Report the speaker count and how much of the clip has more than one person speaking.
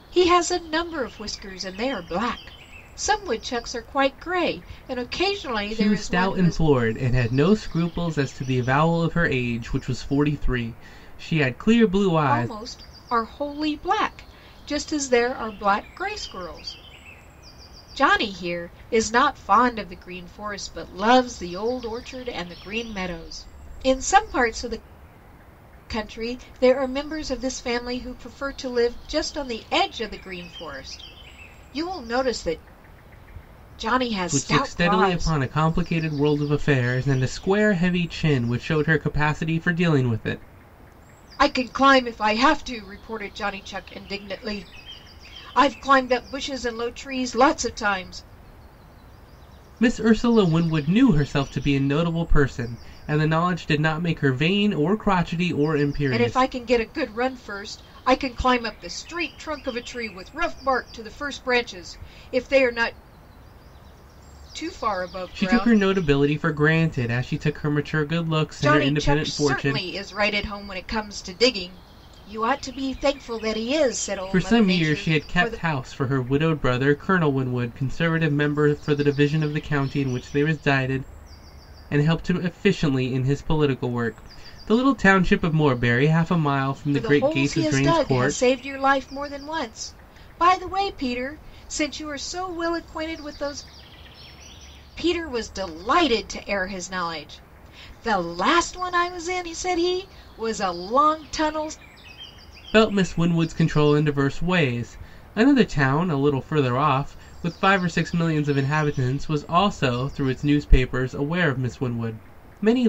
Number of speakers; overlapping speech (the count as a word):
two, about 7%